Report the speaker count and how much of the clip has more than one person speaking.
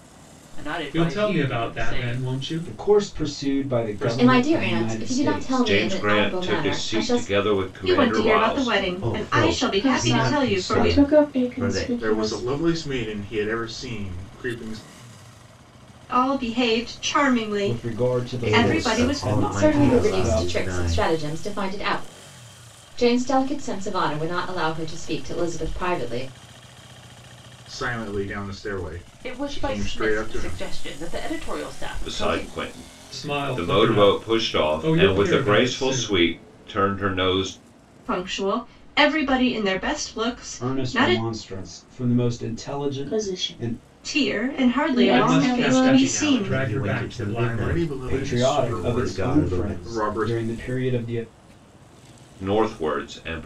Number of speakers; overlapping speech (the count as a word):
nine, about 50%